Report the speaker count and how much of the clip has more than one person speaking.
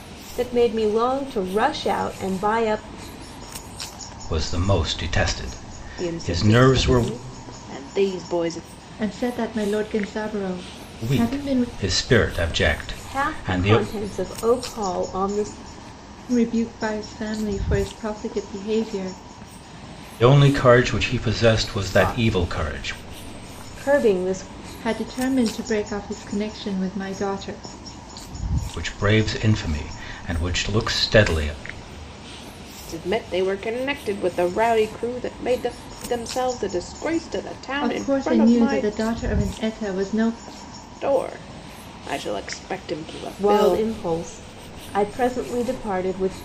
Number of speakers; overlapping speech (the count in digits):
4, about 12%